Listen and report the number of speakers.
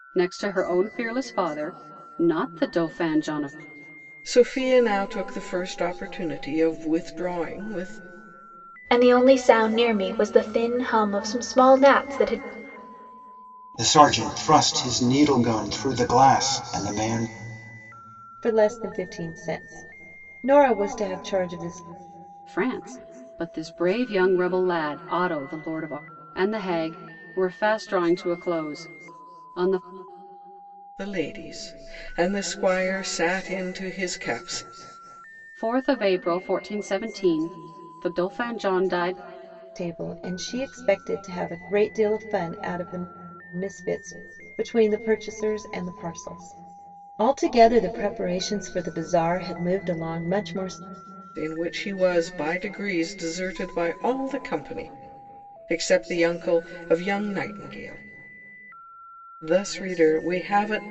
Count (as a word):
five